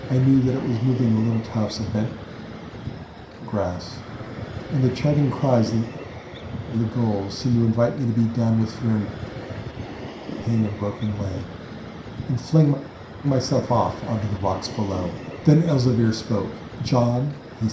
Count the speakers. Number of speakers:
one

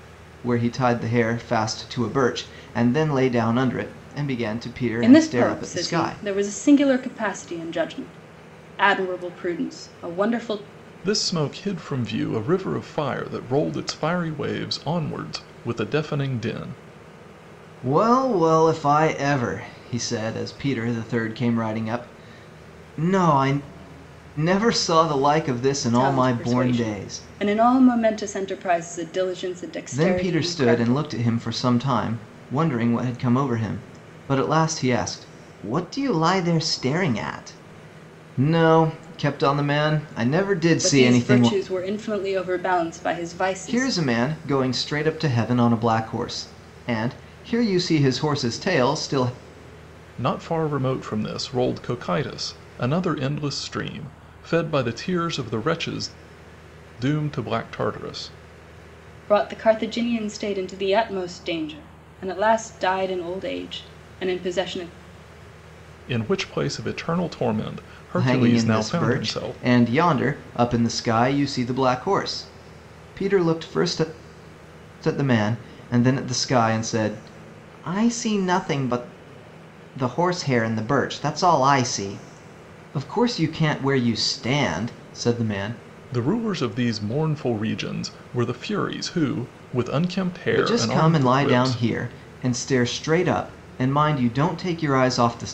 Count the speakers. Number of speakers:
three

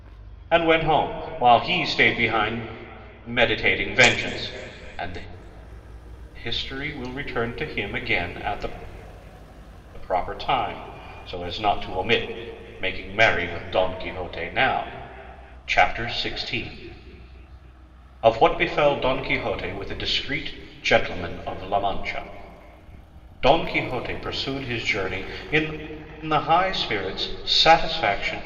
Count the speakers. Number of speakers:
one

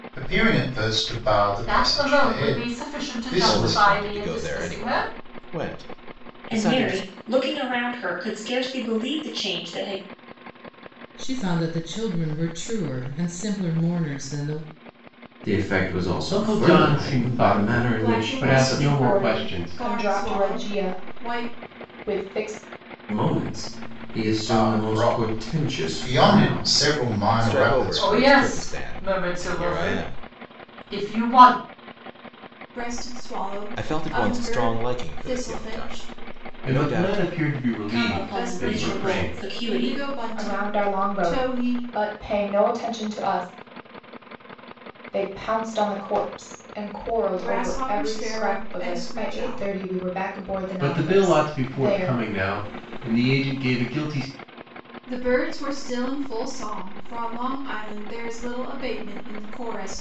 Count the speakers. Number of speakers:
nine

